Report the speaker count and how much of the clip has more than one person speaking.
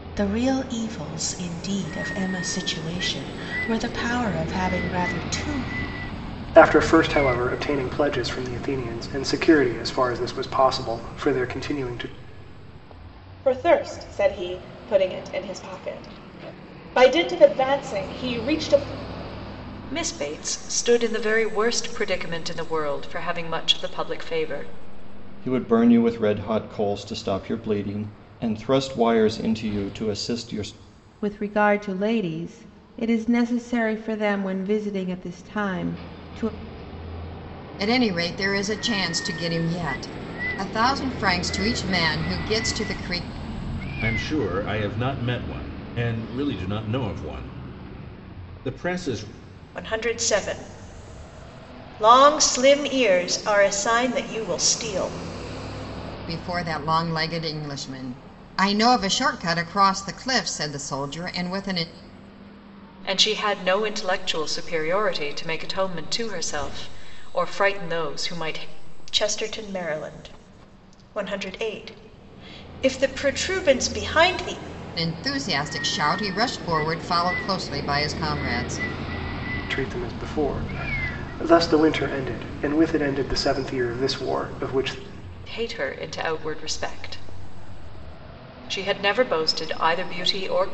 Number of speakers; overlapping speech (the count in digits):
9, no overlap